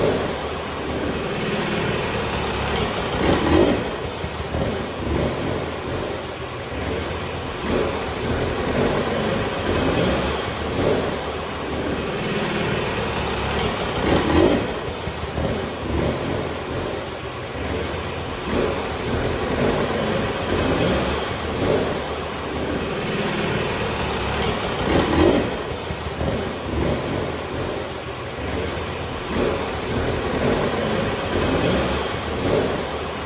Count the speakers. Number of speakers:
0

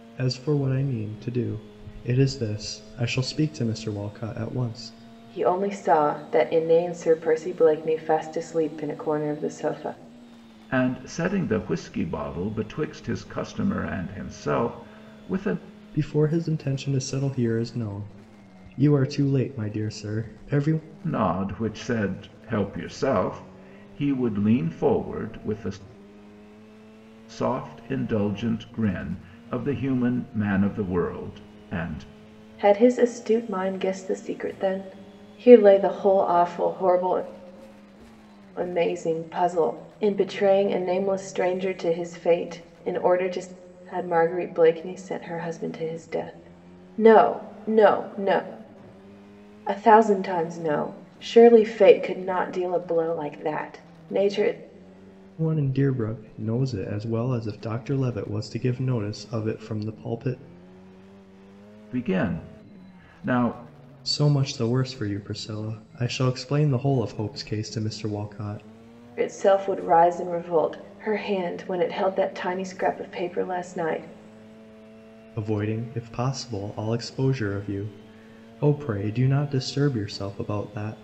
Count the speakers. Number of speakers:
3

